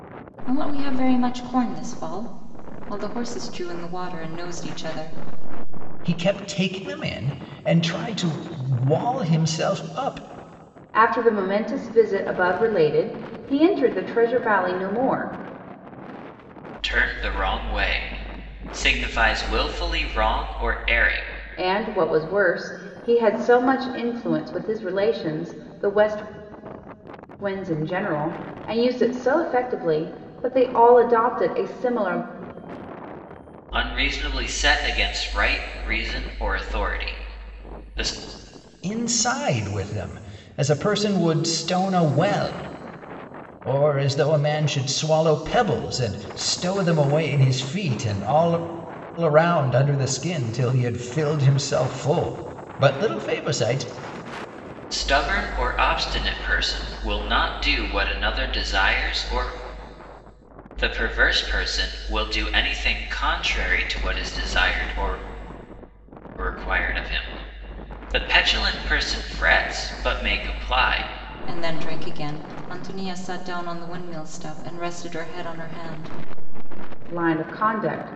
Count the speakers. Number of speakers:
4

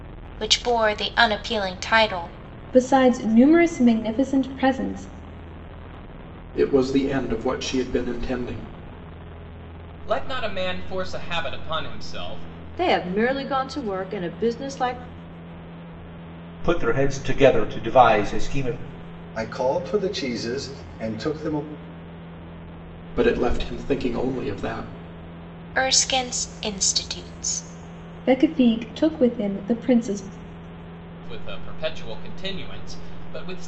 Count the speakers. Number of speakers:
7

